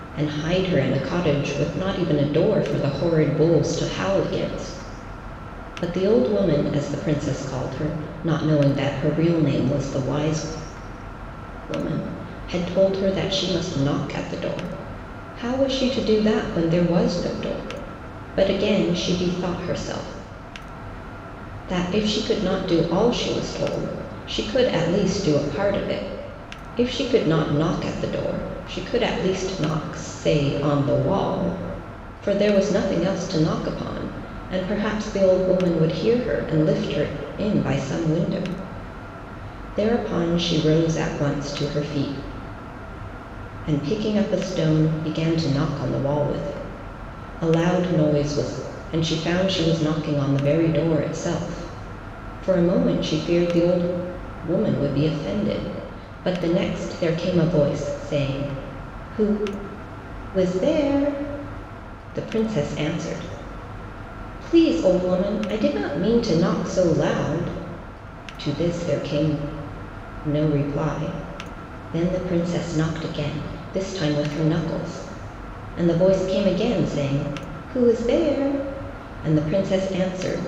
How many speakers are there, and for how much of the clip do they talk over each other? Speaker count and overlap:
one, no overlap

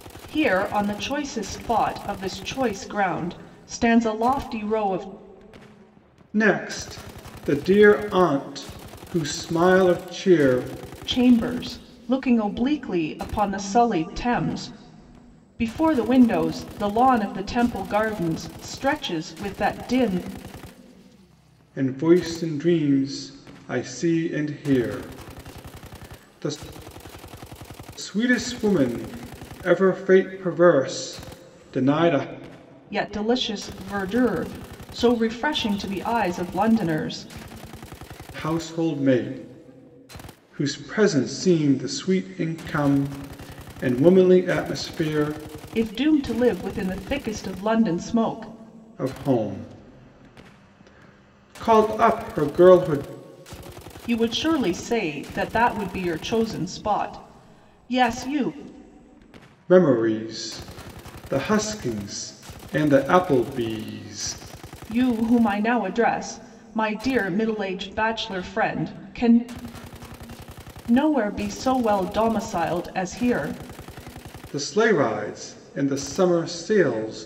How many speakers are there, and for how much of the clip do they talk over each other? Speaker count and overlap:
two, no overlap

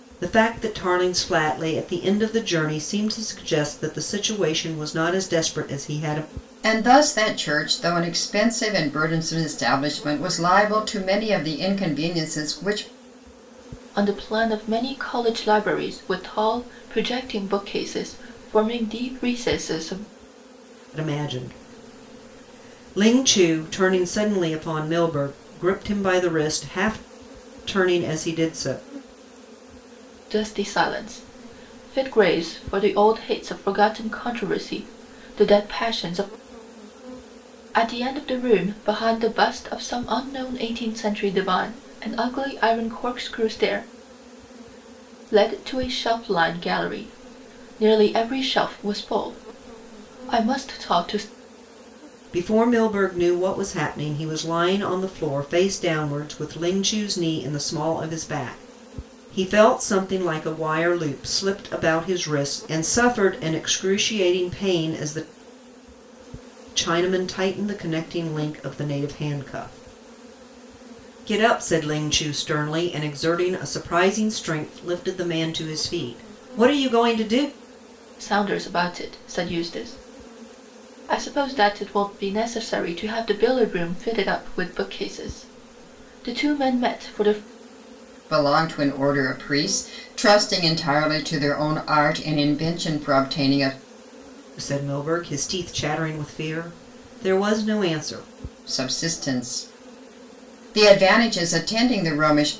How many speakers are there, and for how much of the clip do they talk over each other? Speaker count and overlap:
three, no overlap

